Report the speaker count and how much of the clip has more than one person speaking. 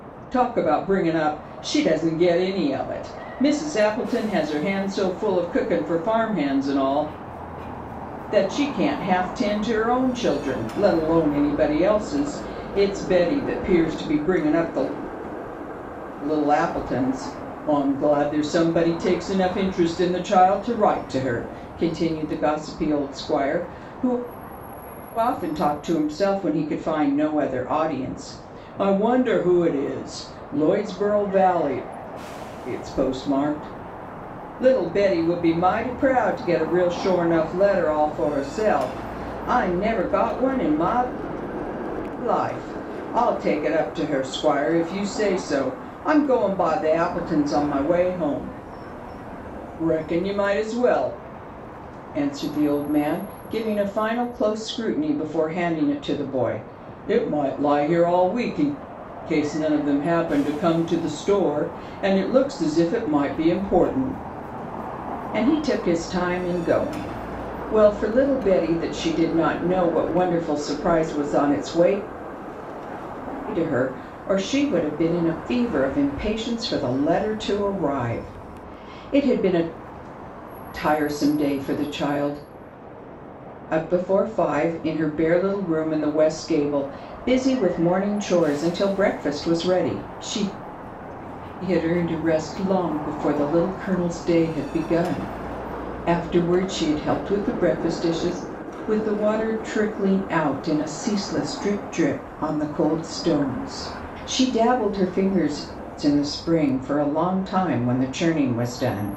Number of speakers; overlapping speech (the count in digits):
1, no overlap